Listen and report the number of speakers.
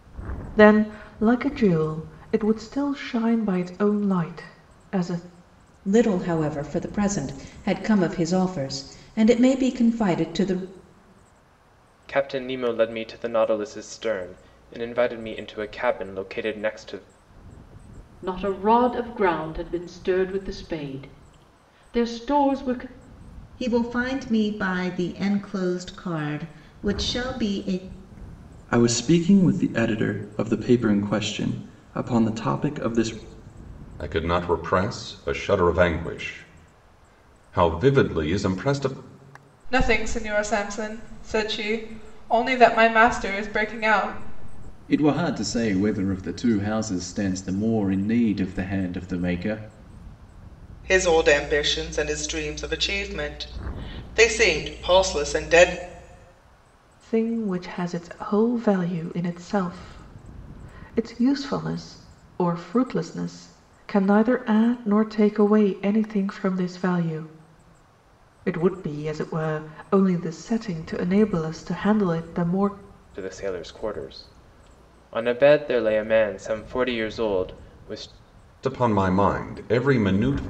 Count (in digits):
10